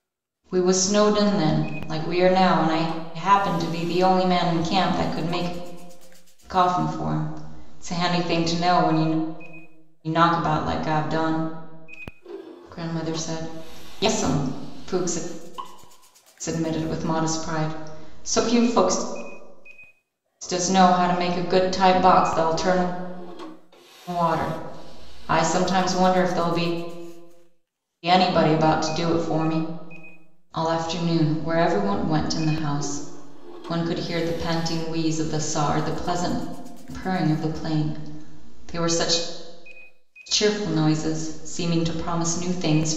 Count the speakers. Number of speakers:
one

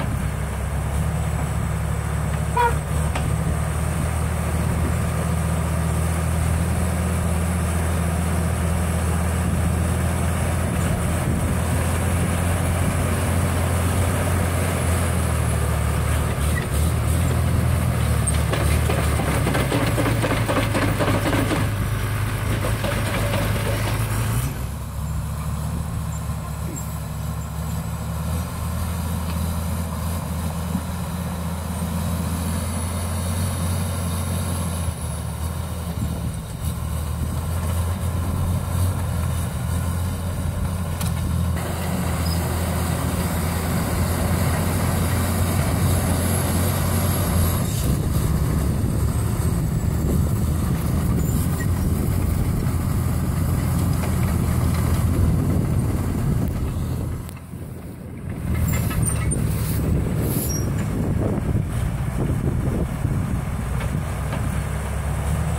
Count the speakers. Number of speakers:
zero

